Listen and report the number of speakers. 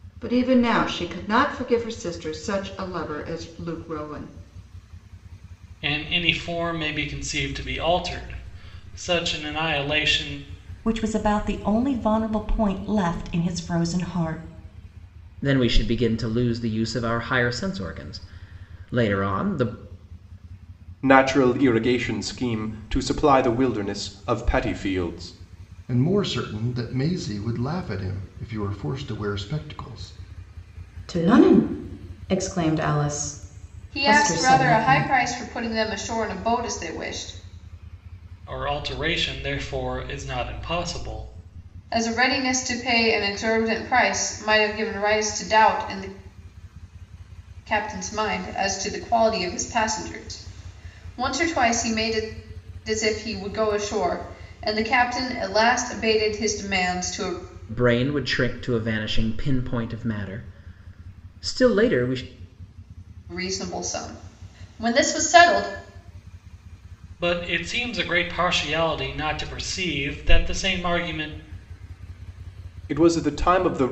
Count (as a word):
eight